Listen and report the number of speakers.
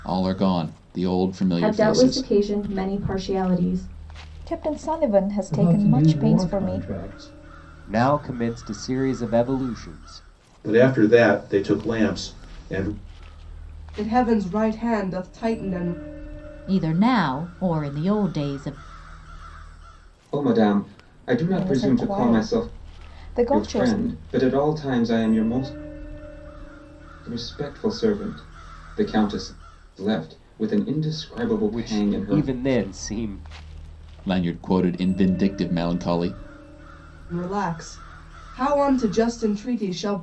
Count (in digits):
9